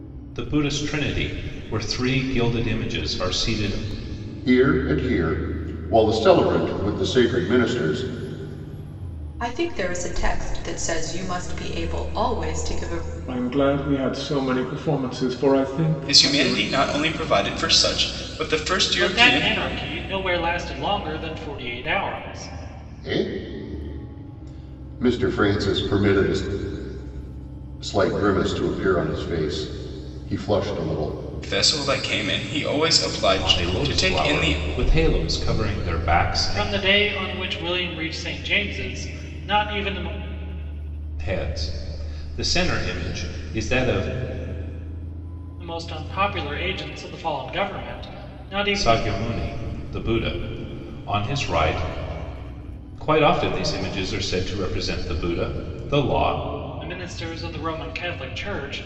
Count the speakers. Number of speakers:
six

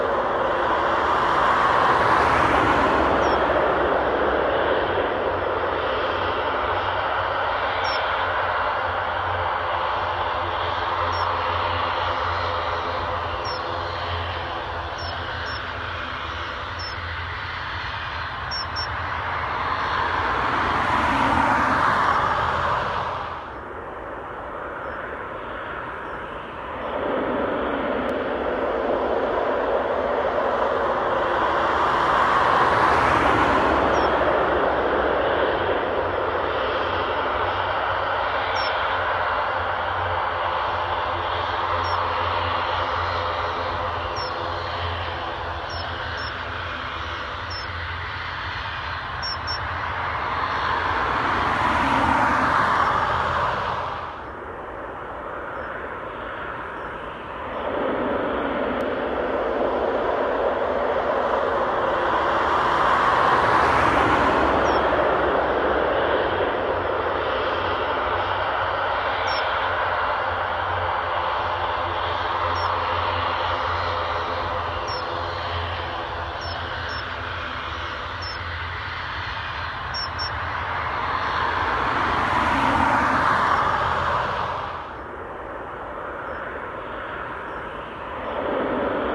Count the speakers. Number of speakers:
zero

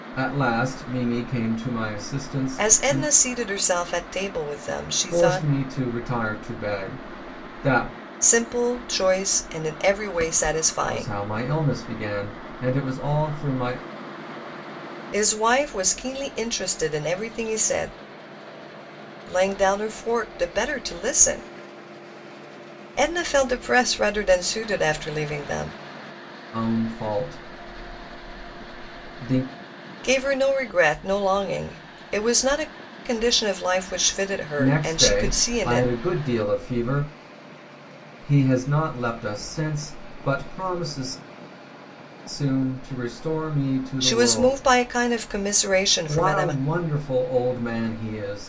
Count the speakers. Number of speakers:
two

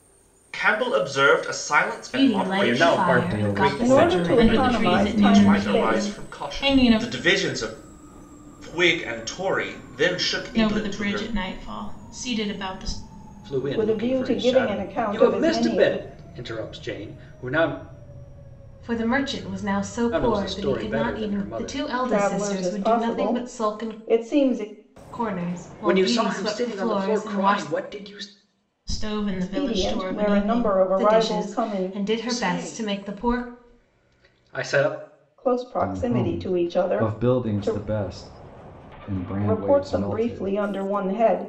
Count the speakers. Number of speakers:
six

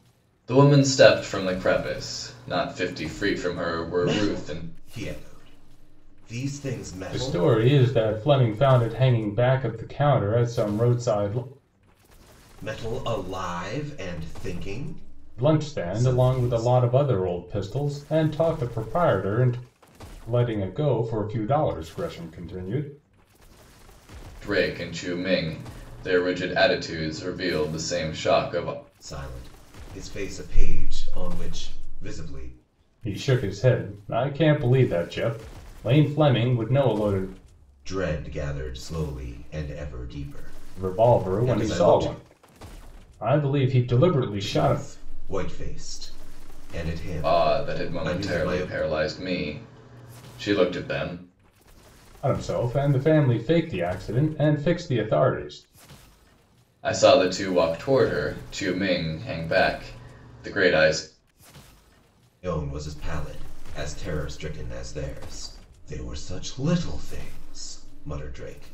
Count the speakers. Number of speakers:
three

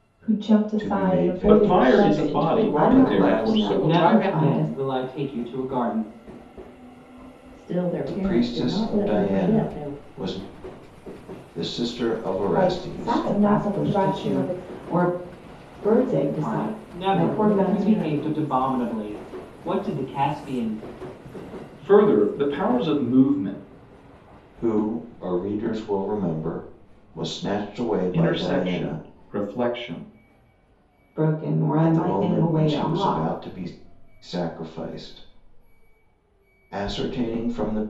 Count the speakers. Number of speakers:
seven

